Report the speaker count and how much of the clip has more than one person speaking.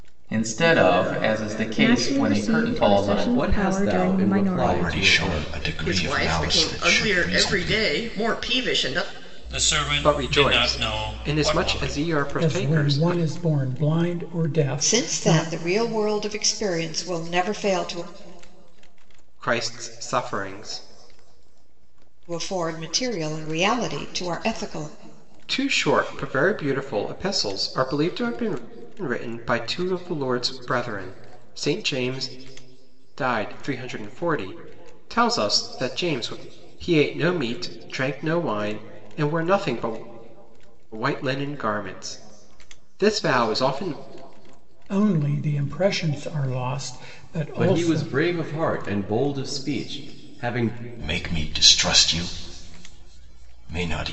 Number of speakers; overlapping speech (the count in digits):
9, about 19%